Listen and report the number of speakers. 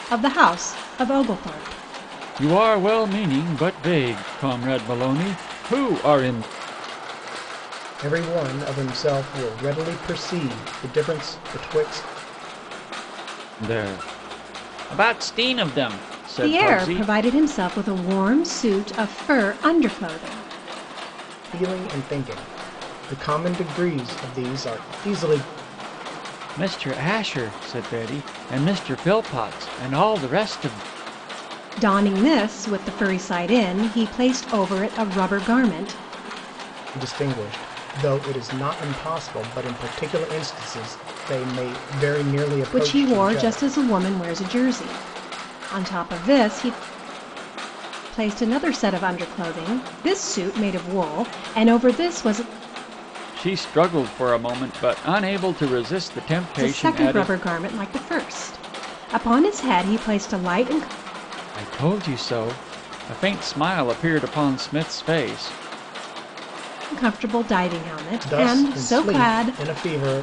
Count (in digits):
3